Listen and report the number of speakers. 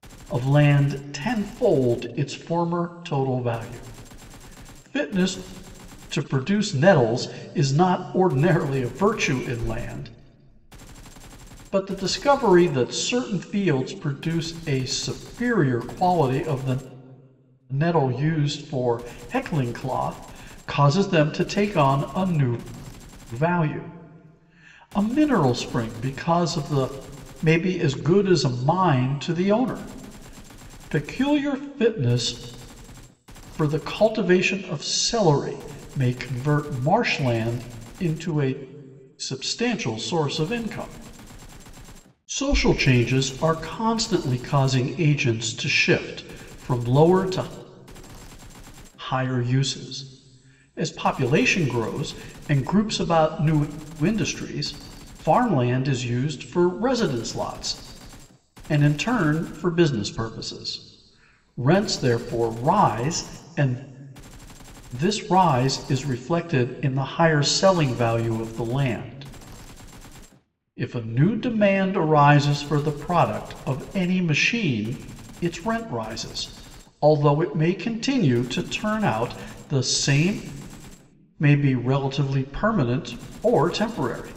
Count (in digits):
1